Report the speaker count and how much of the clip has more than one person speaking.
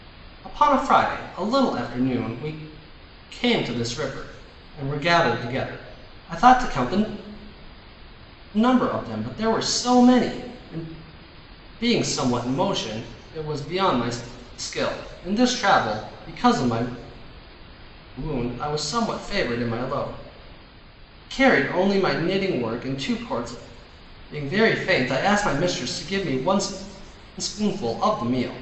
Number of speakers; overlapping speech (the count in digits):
1, no overlap